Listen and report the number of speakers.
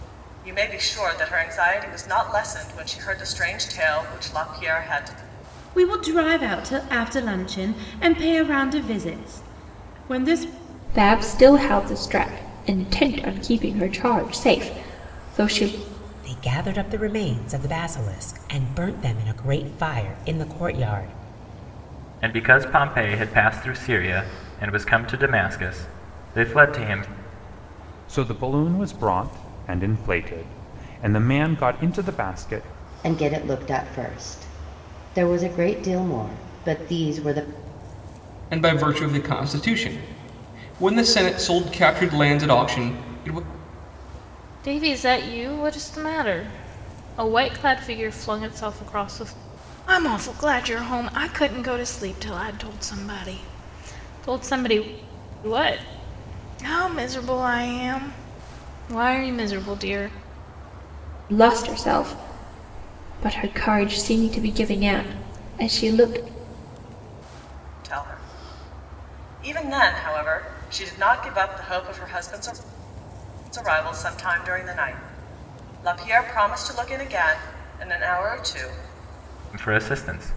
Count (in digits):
9